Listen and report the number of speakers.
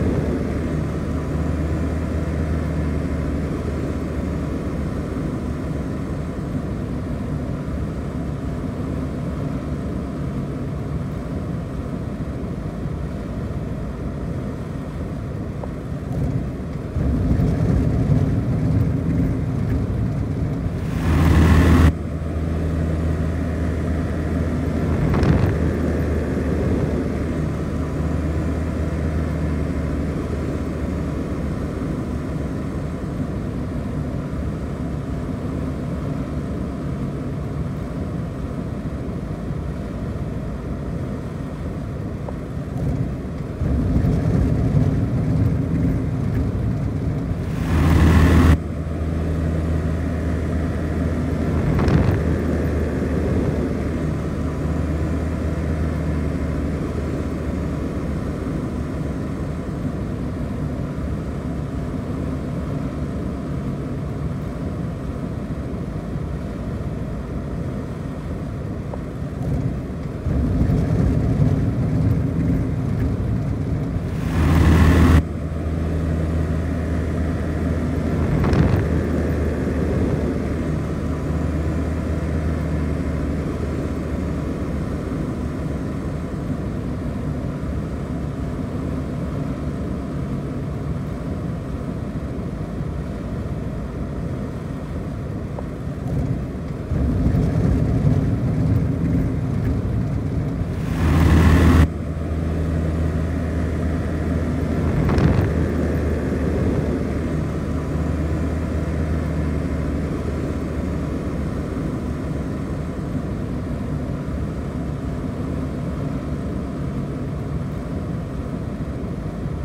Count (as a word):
zero